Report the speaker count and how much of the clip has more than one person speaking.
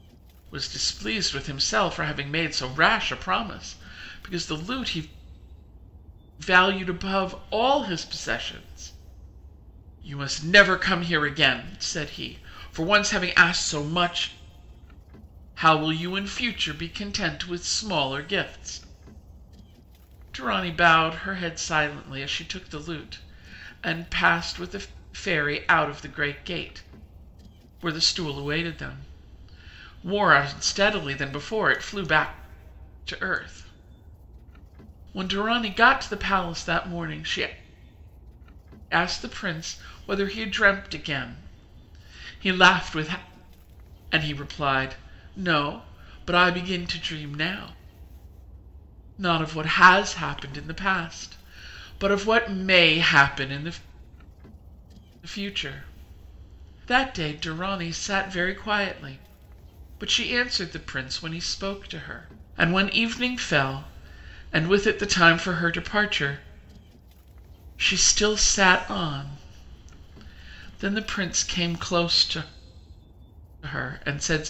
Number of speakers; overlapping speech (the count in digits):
1, no overlap